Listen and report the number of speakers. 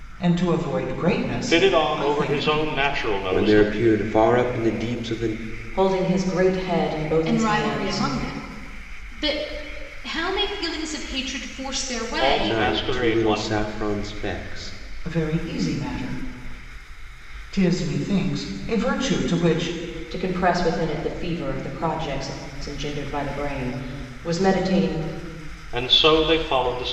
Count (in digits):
5